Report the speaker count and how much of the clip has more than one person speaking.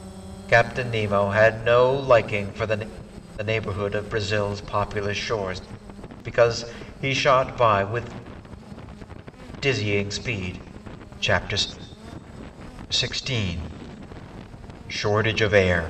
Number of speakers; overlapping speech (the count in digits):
1, no overlap